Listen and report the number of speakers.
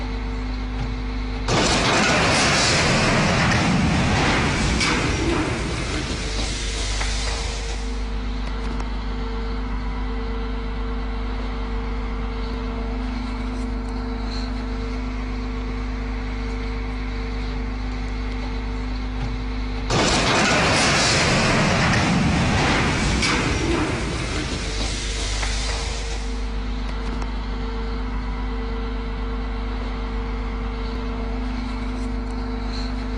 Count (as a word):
zero